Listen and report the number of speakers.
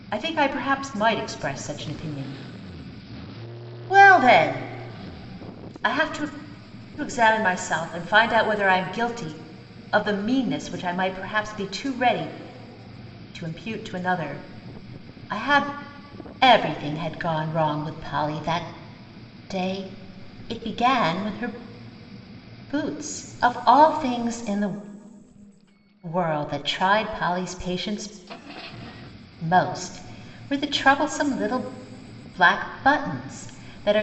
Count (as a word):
one